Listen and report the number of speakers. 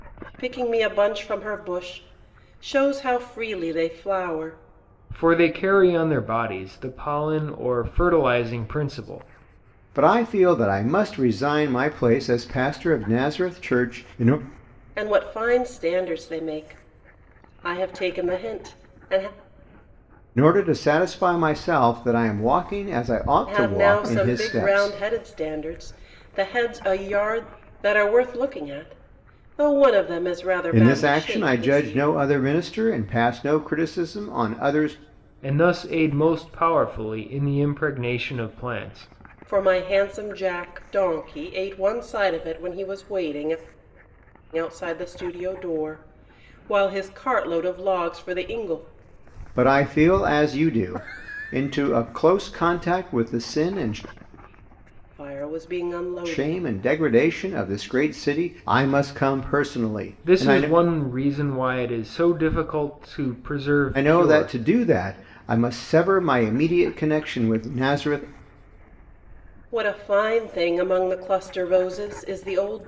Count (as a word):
three